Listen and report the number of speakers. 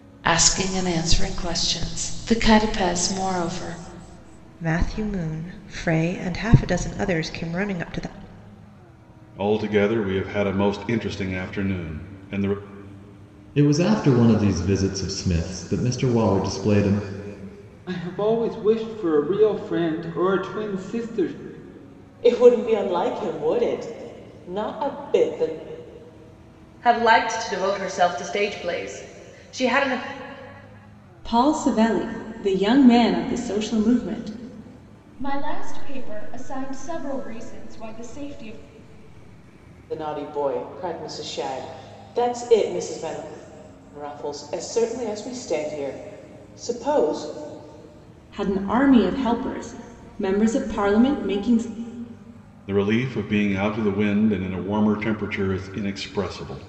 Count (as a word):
nine